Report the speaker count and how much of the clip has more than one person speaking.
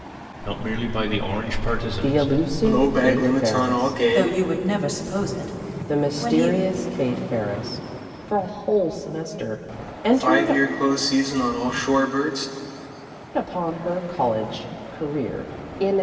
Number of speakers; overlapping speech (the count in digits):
4, about 22%